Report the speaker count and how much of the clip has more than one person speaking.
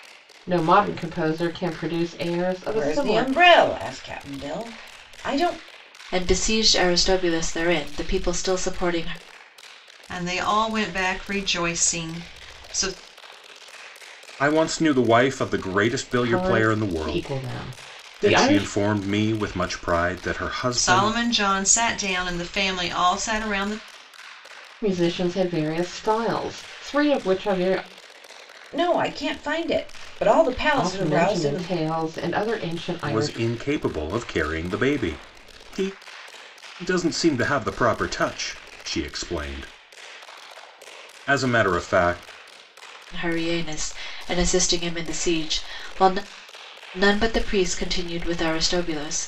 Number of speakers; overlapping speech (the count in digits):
5, about 8%